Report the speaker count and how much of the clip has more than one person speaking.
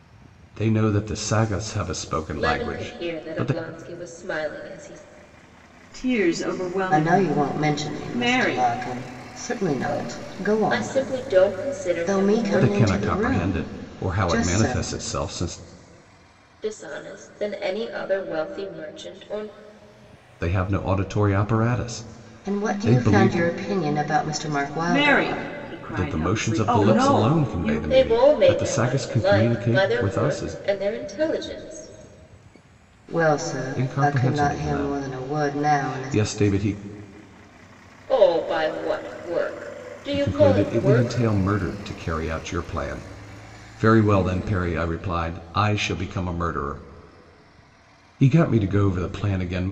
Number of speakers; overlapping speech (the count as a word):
four, about 34%